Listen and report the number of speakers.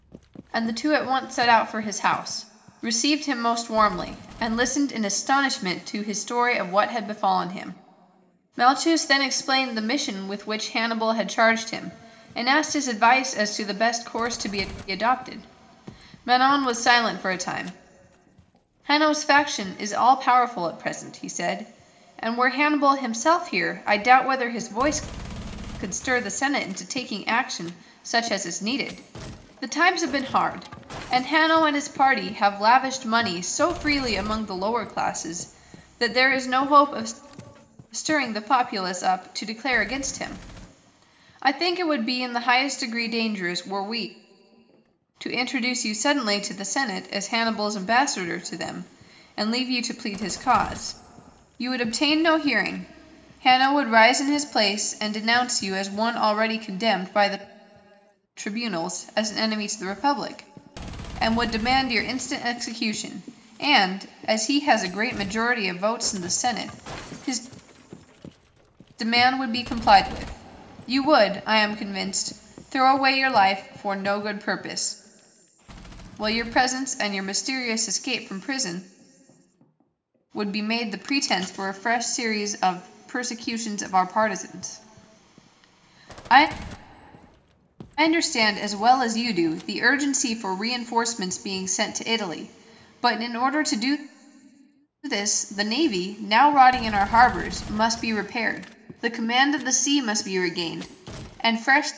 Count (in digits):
1